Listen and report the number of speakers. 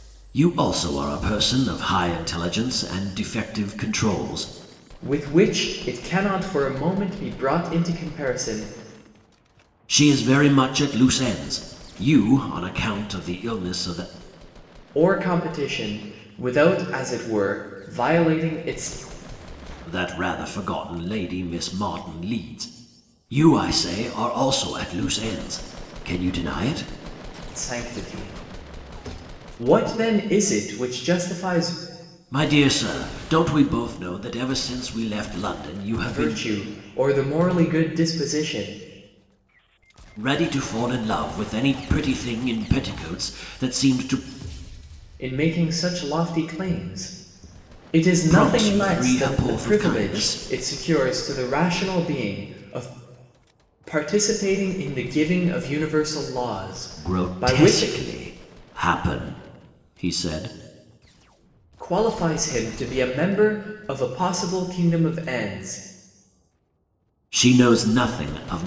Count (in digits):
2